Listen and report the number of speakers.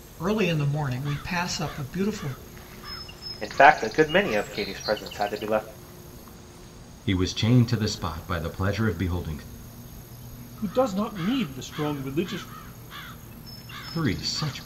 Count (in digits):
4